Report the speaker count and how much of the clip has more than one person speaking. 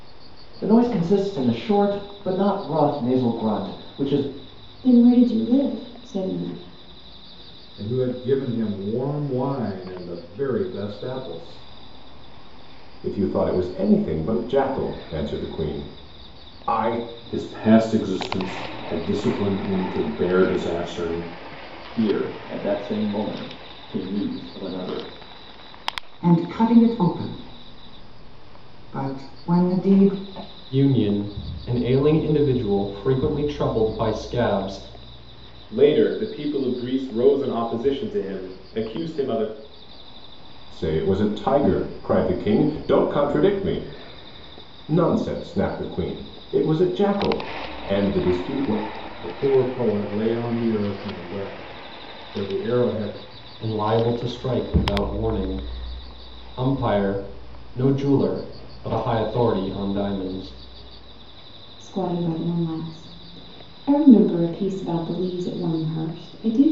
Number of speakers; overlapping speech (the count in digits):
9, no overlap